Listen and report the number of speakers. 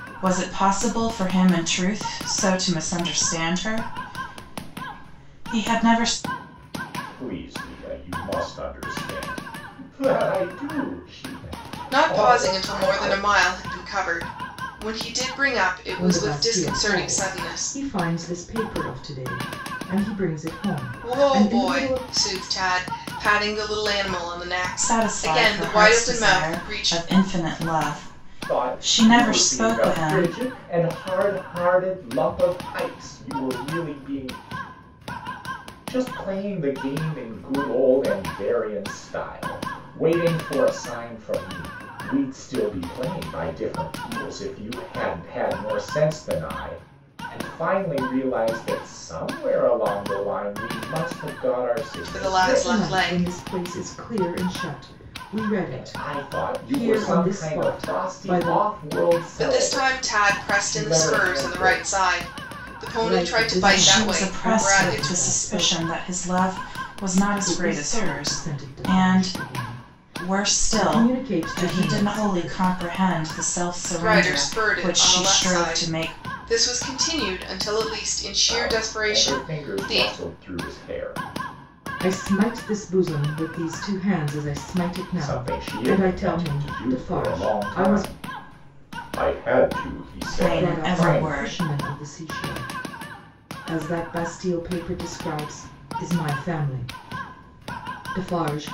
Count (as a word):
four